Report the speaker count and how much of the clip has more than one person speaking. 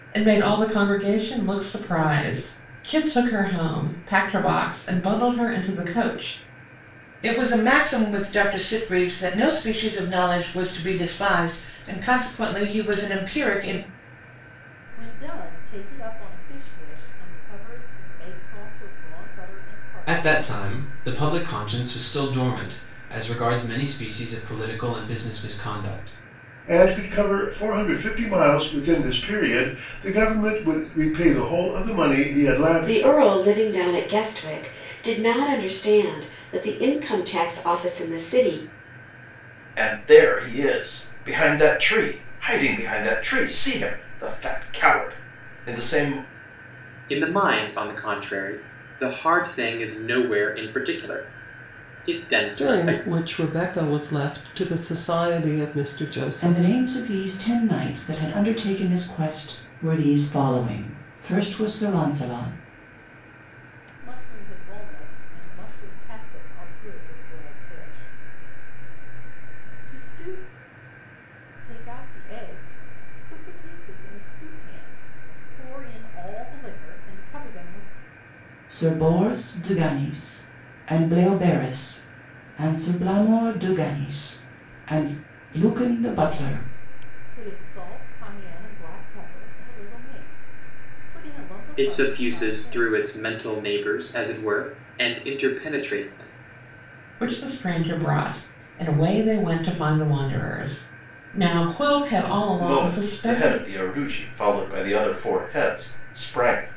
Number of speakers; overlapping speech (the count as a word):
ten, about 5%